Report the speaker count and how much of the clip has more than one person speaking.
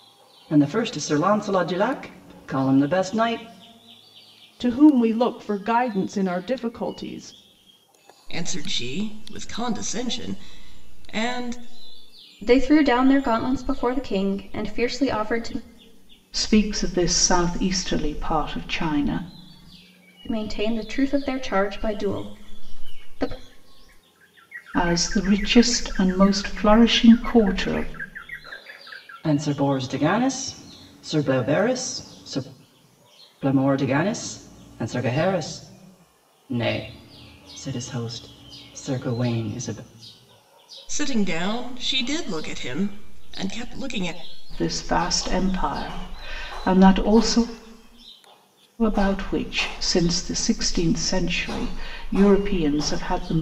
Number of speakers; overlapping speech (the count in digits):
5, no overlap